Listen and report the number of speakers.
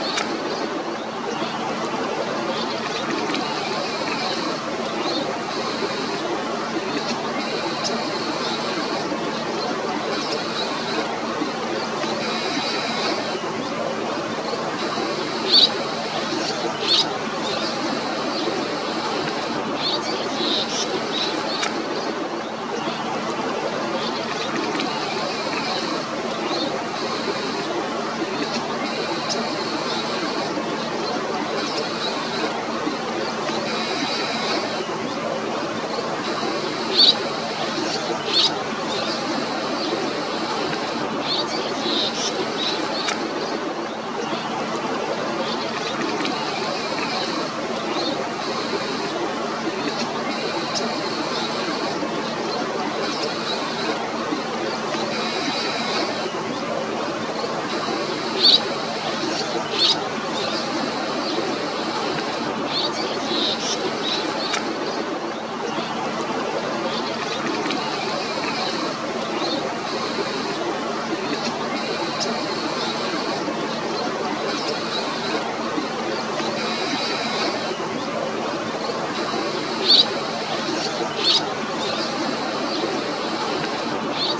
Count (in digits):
0